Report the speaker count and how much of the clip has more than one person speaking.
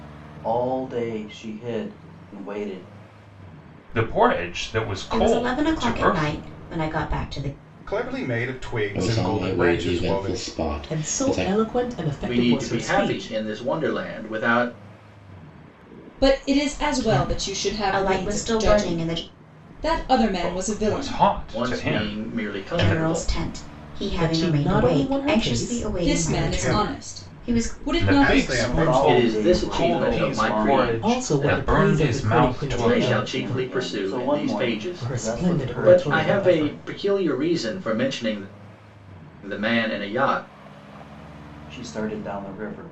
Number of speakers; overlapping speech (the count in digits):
8, about 52%